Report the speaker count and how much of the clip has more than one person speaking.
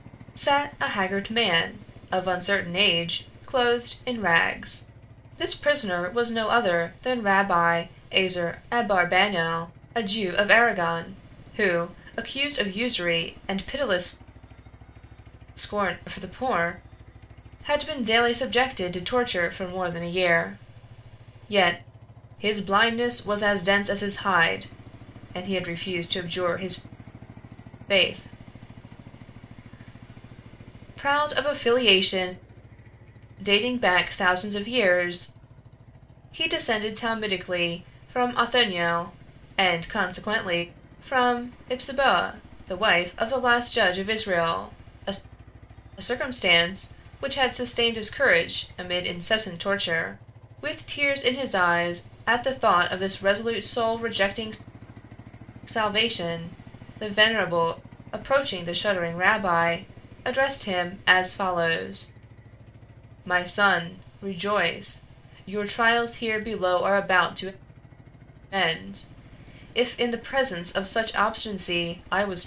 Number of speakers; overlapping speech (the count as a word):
one, no overlap